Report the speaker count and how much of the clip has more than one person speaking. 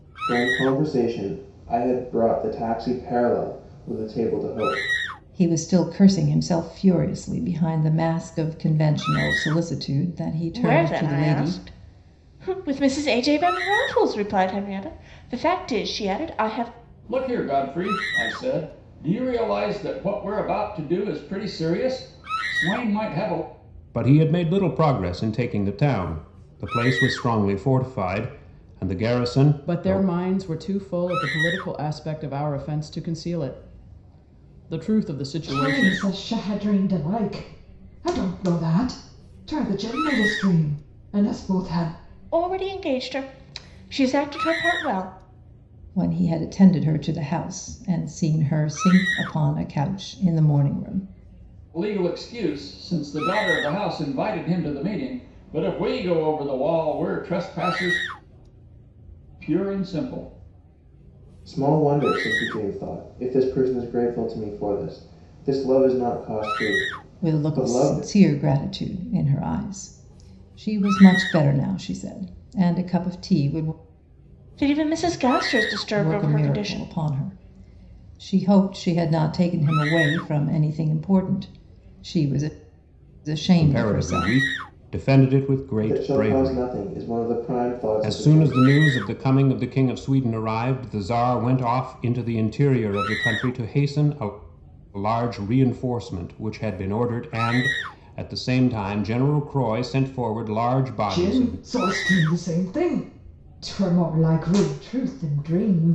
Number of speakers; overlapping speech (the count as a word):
seven, about 7%